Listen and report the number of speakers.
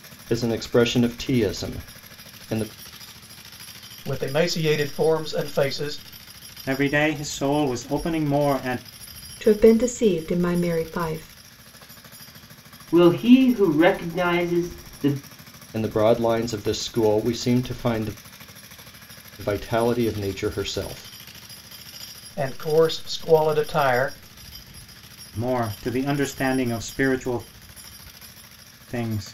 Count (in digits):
5